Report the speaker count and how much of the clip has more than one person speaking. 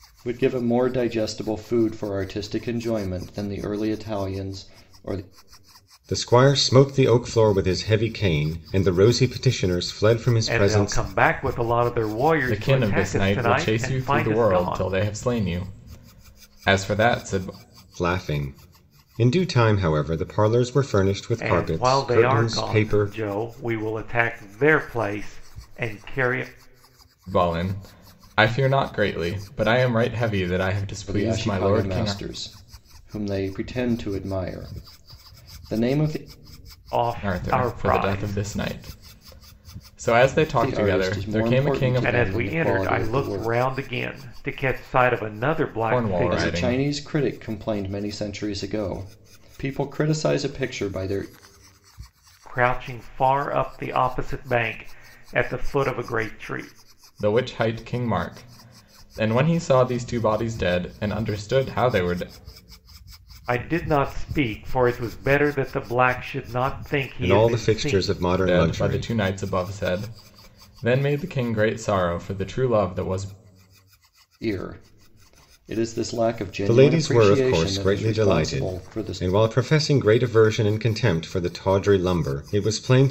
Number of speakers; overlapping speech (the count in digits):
4, about 19%